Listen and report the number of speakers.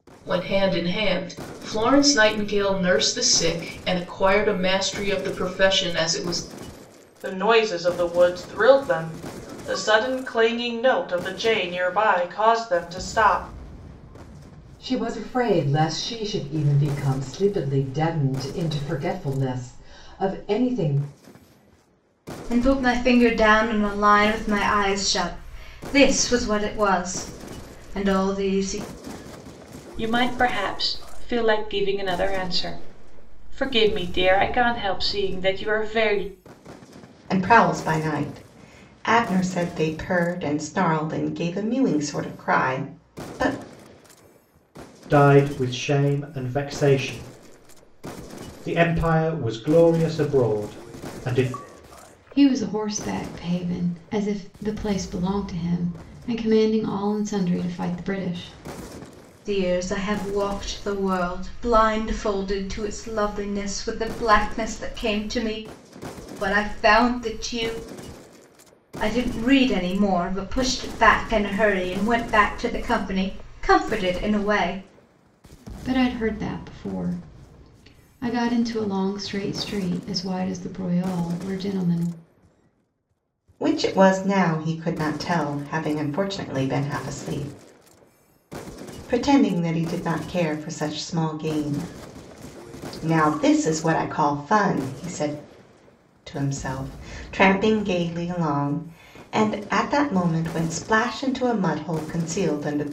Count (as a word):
eight